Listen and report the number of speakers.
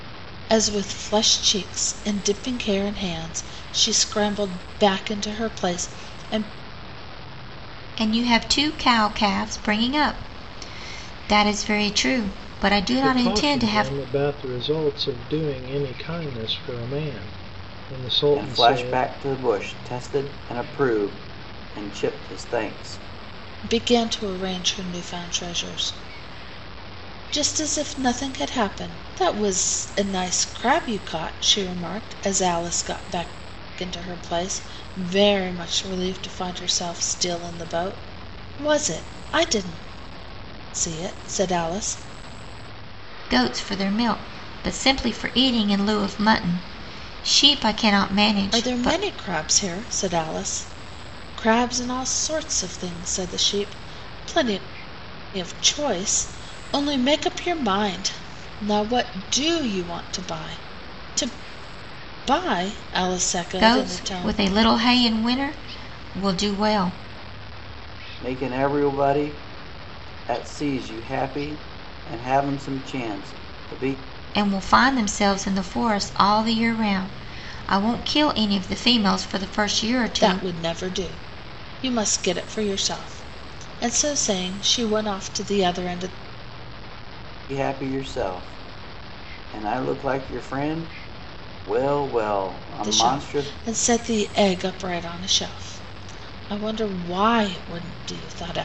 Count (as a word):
four